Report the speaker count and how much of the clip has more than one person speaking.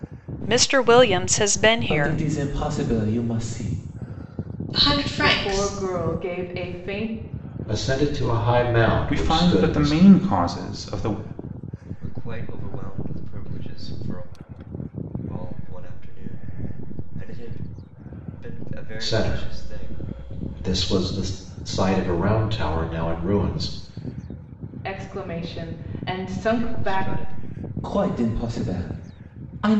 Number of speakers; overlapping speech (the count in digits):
7, about 12%